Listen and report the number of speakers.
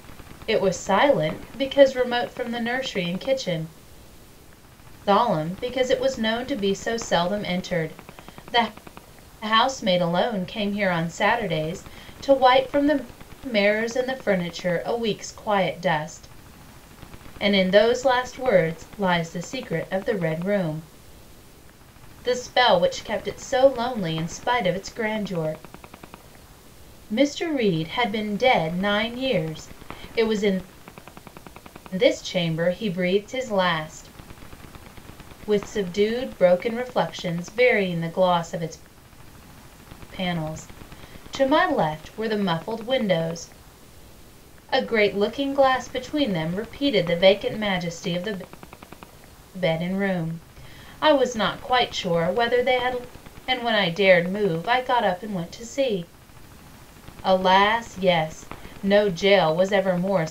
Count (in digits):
1